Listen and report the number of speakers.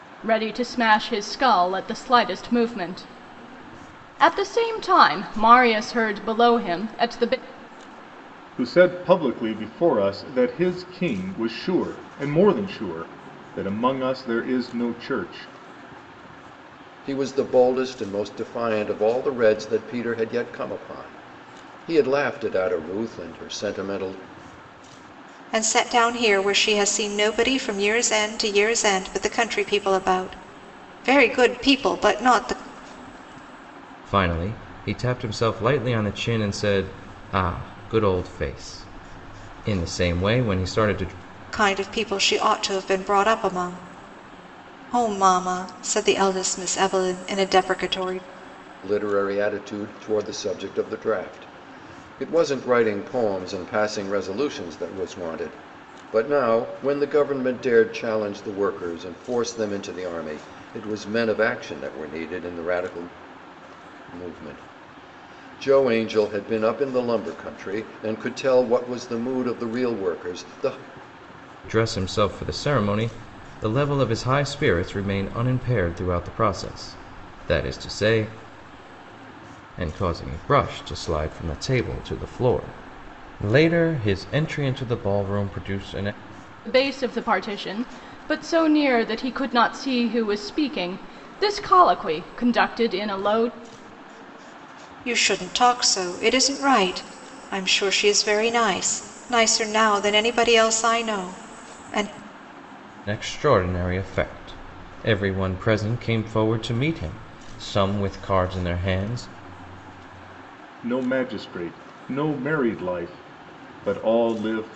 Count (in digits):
5